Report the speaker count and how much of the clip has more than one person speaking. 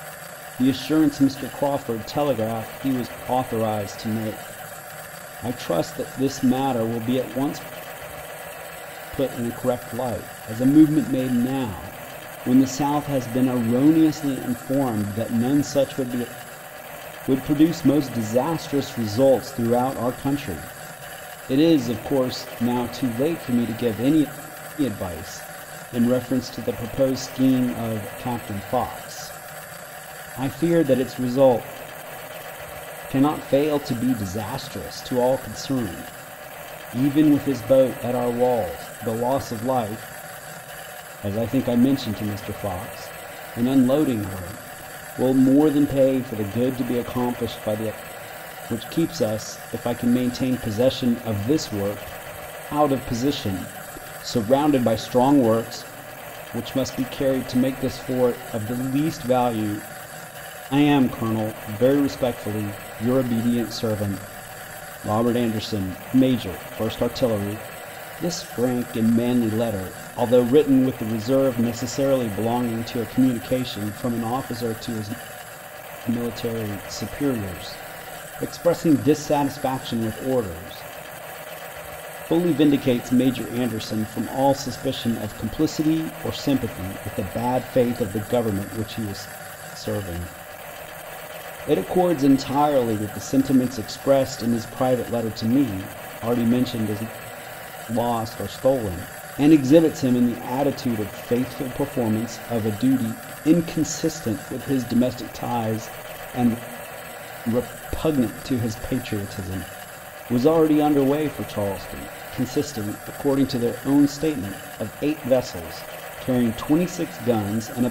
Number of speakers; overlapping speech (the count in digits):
1, no overlap